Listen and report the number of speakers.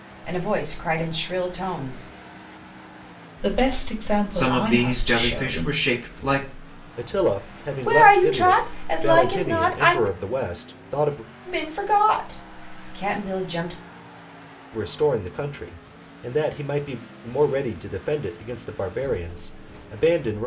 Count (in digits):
4